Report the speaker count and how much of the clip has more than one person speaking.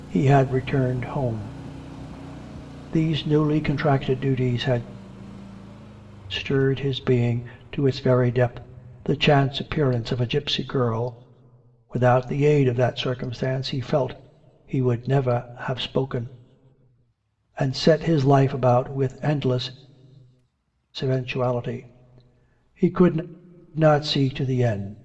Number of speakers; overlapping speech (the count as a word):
one, no overlap